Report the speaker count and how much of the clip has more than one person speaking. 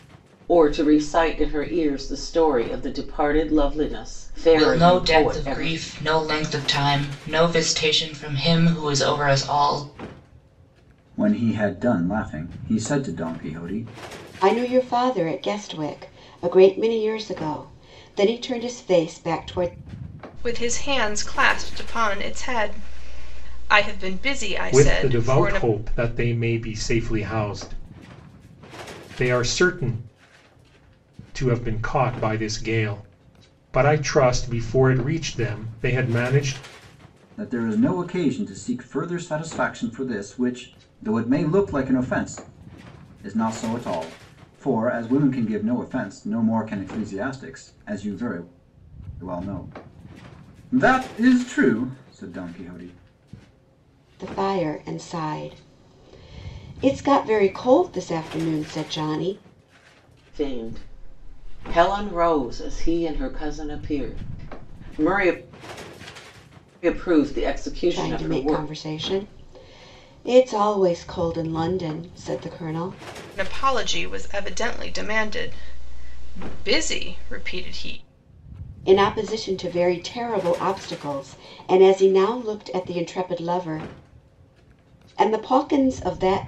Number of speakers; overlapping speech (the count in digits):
6, about 4%